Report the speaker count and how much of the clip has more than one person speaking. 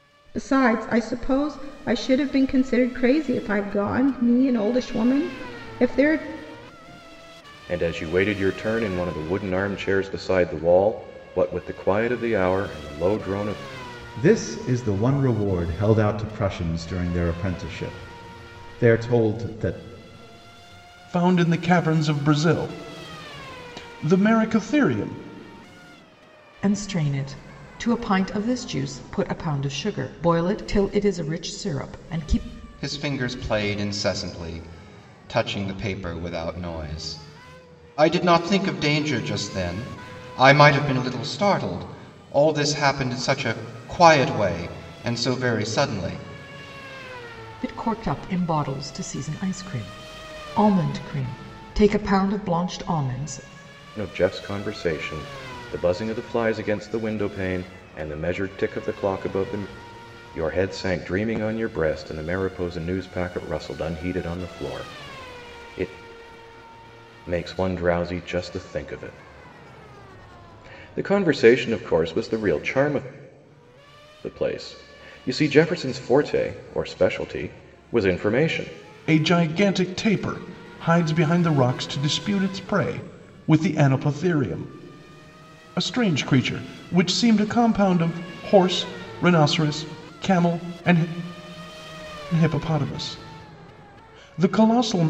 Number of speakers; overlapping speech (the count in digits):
6, no overlap